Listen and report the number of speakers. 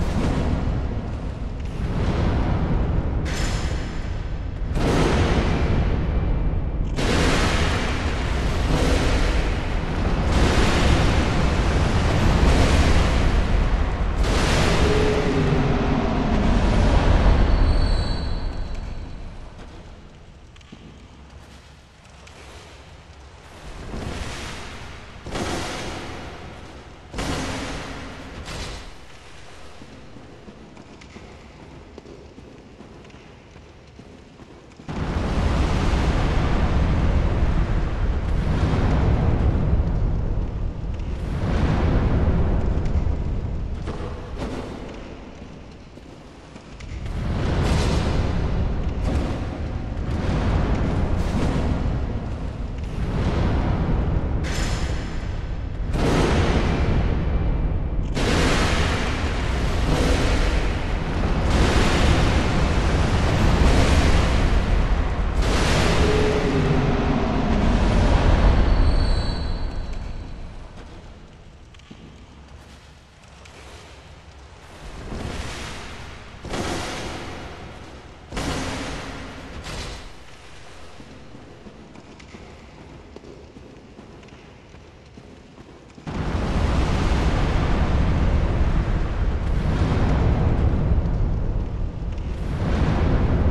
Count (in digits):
0